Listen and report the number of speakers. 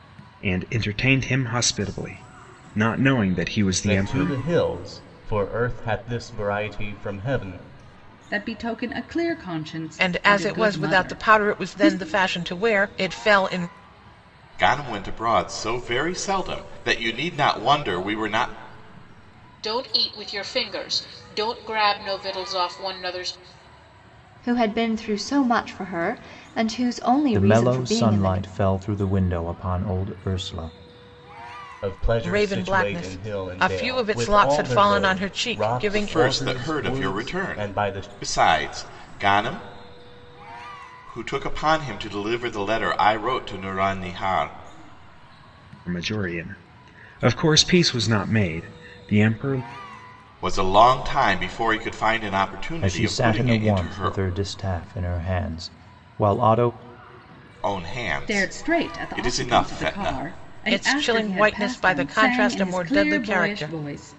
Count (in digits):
8